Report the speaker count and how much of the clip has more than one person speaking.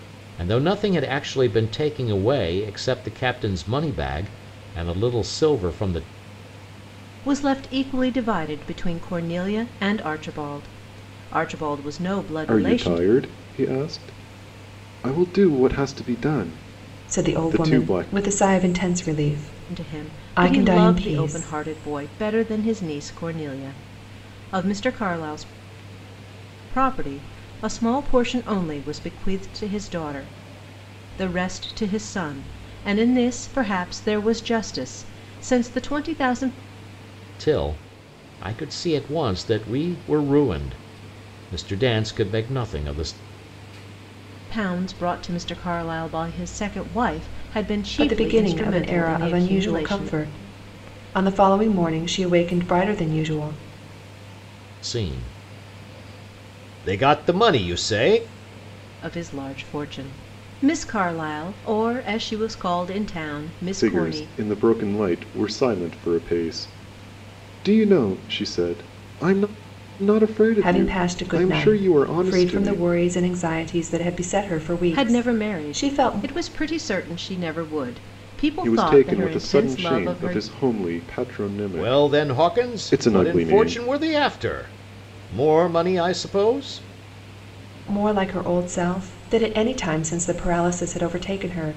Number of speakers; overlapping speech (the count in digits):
4, about 16%